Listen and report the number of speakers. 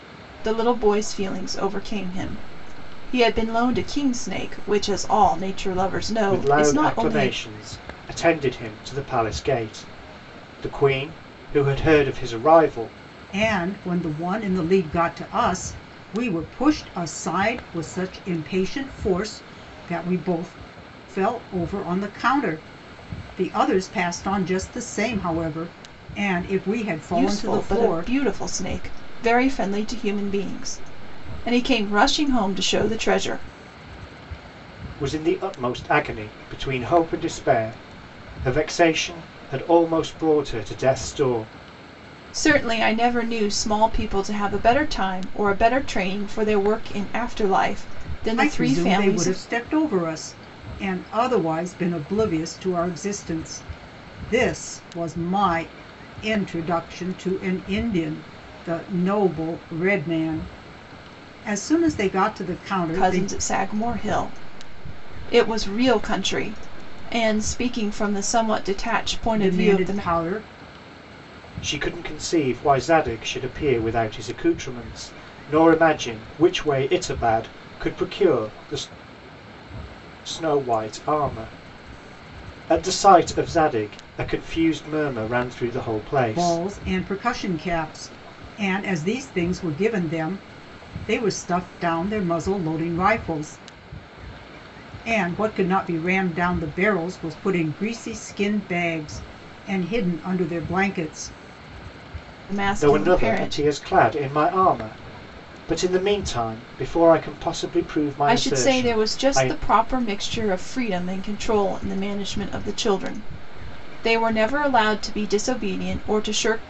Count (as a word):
three